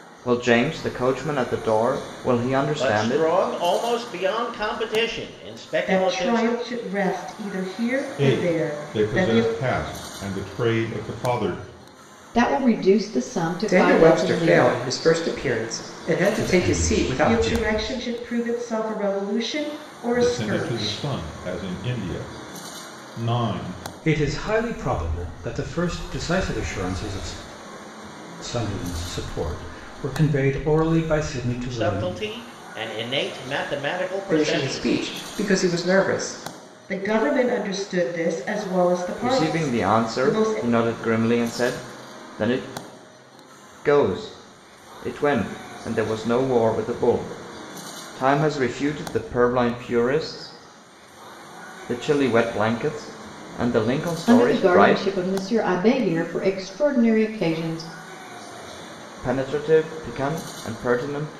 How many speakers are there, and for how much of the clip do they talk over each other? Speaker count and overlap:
seven, about 16%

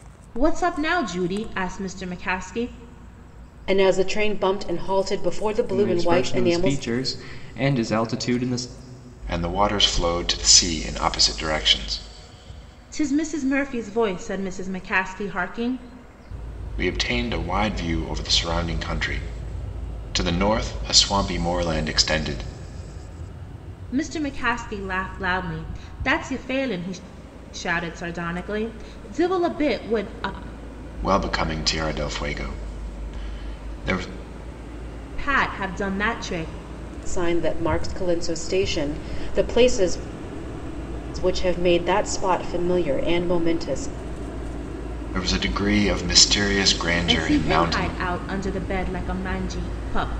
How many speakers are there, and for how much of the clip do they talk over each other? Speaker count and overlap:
four, about 4%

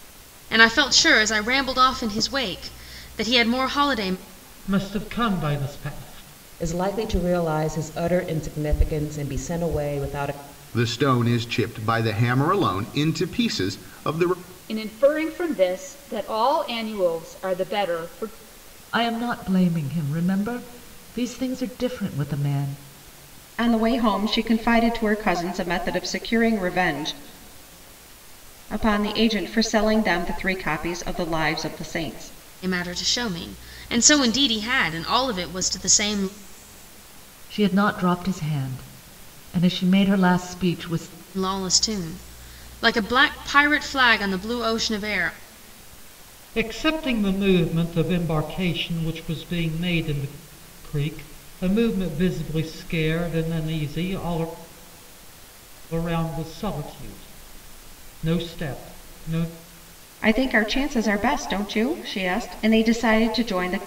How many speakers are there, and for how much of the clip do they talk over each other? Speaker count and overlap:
seven, no overlap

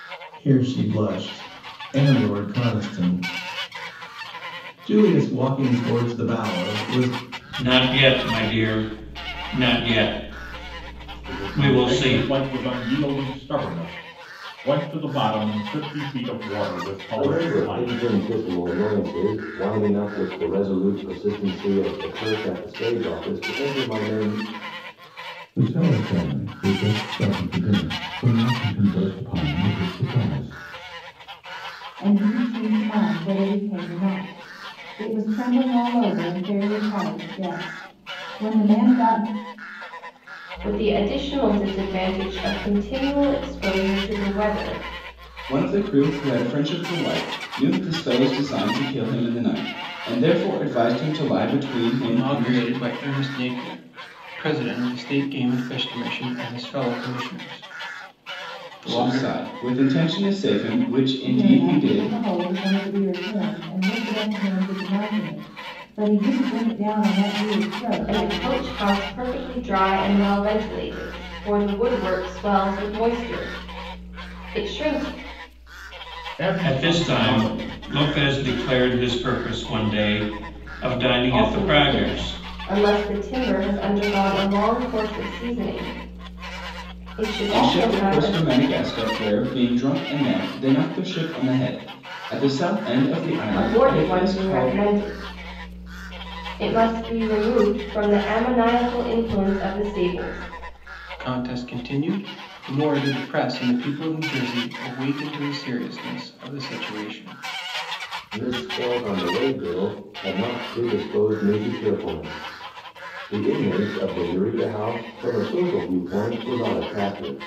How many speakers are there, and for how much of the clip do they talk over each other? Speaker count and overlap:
nine, about 8%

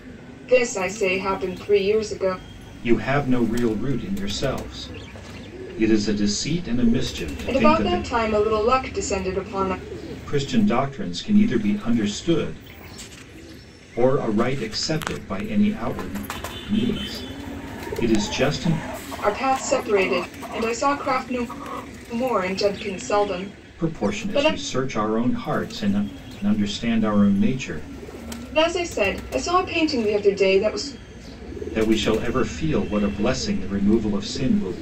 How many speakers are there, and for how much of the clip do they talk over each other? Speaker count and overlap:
two, about 4%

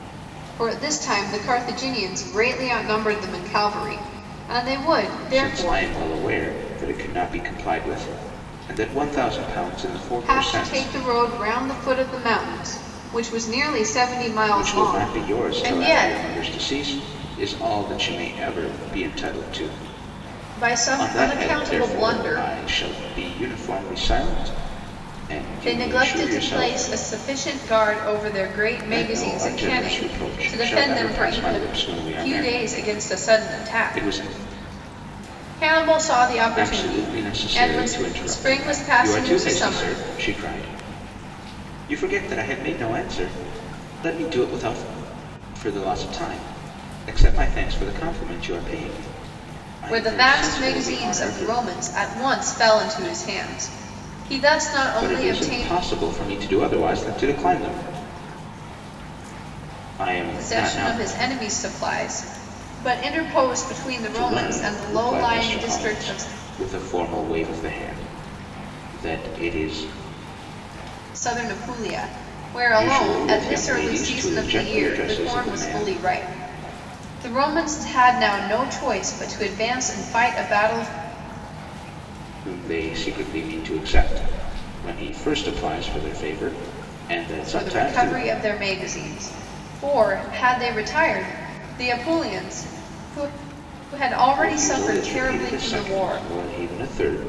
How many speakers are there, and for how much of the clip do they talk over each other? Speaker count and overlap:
two, about 26%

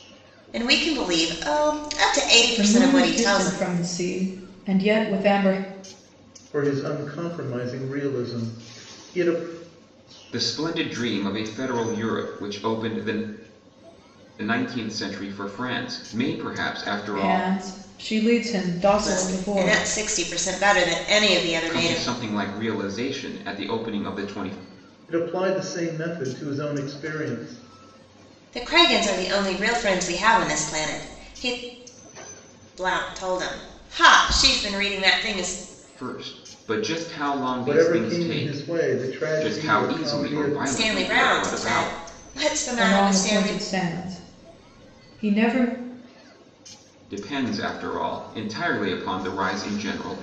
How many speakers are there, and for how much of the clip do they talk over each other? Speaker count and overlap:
four, about 14%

